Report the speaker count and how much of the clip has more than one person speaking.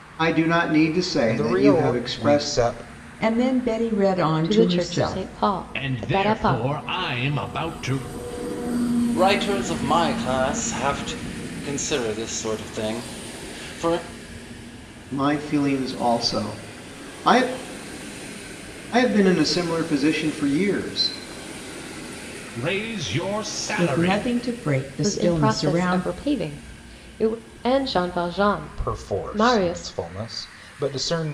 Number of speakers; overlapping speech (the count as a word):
six, about 20%